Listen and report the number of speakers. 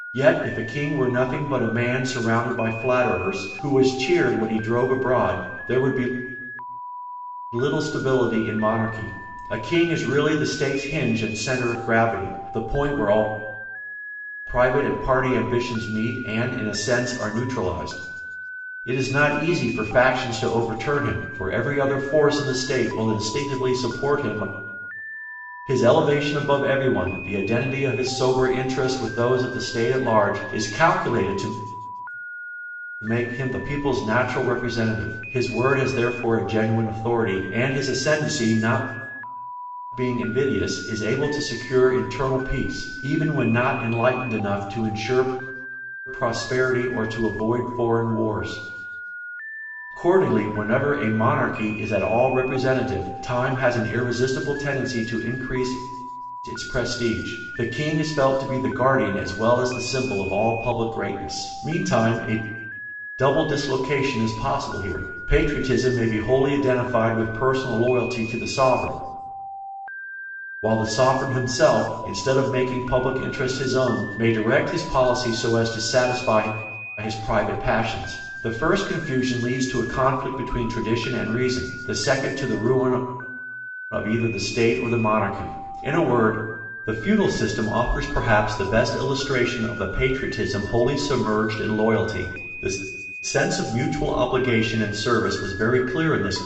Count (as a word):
one